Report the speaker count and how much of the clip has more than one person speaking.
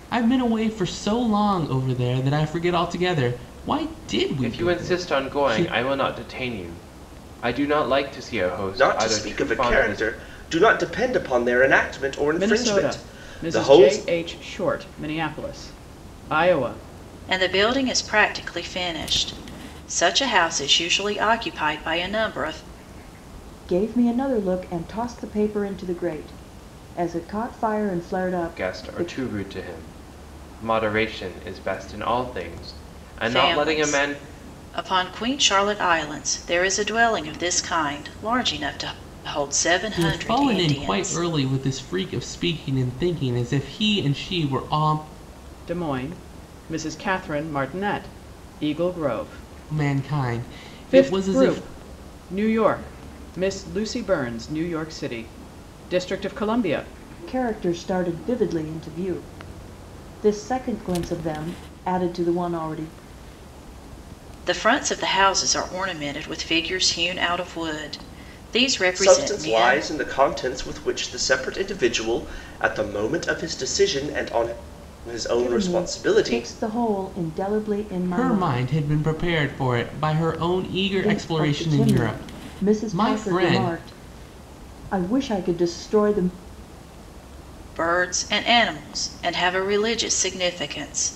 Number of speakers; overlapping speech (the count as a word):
six, about 16%